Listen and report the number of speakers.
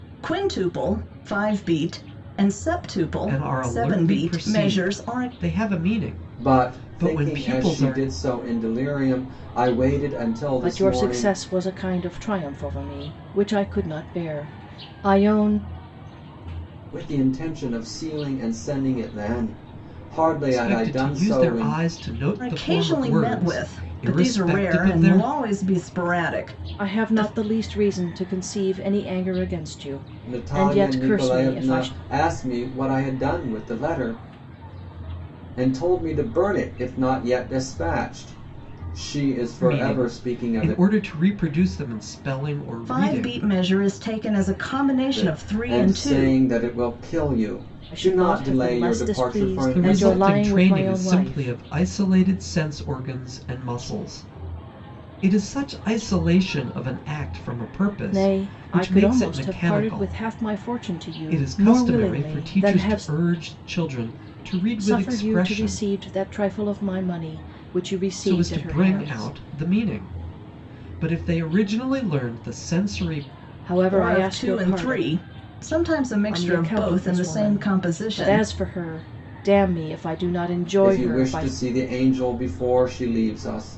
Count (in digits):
4